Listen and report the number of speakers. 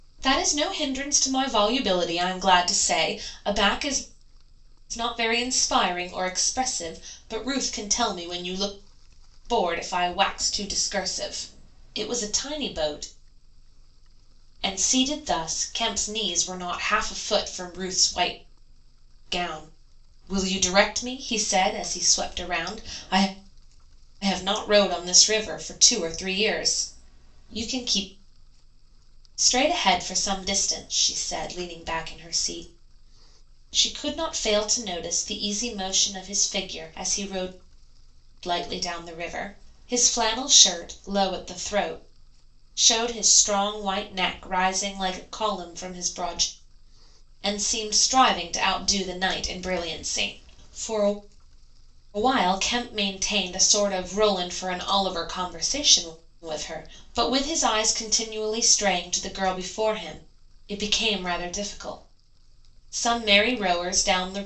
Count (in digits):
1